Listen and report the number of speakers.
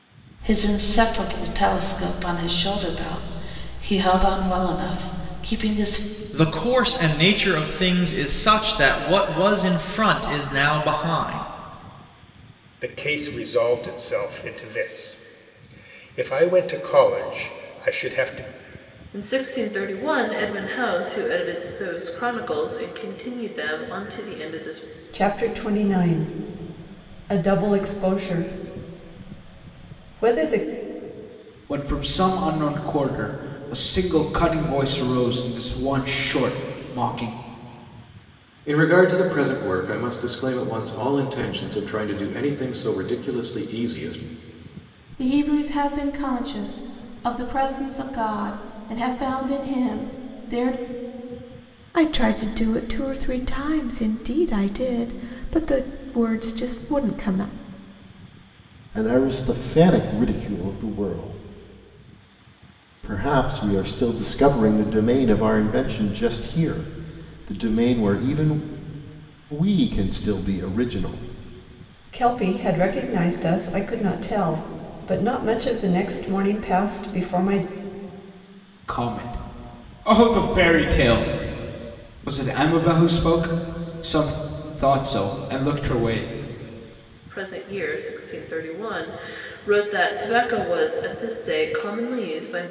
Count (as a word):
ten